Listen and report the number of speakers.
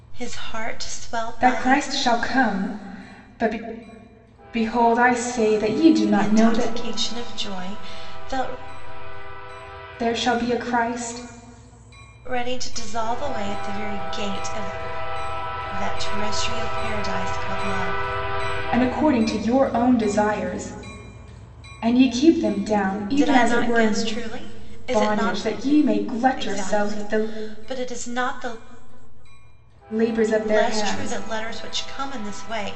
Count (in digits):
2